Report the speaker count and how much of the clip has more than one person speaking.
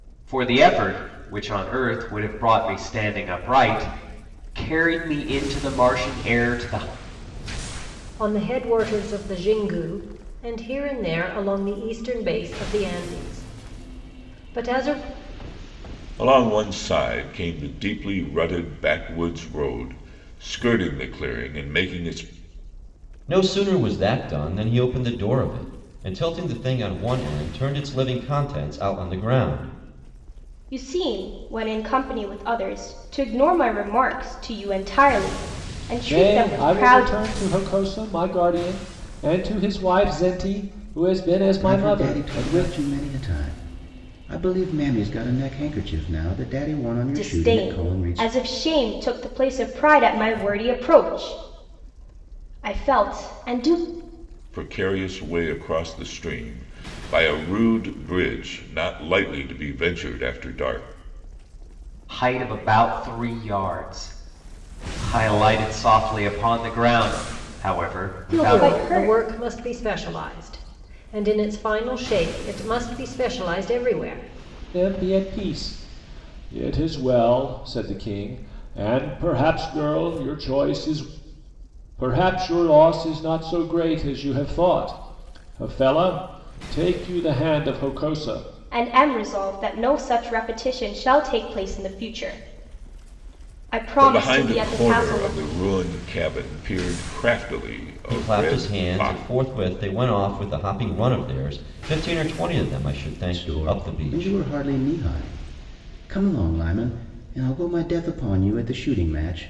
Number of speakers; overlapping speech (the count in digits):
7, about 8%